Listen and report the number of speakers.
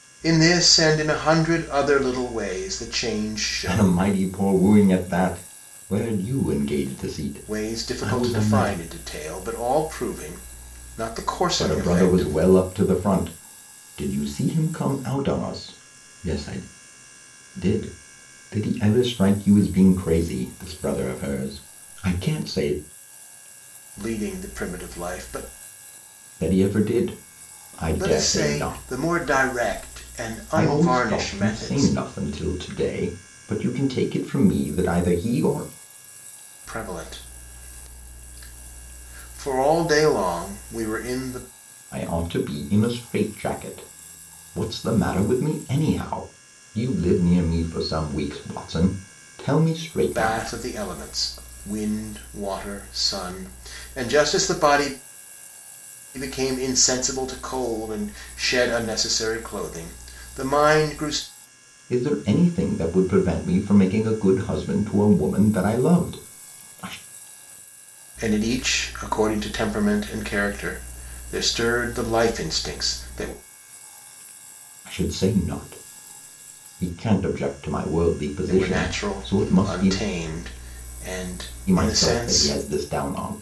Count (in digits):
2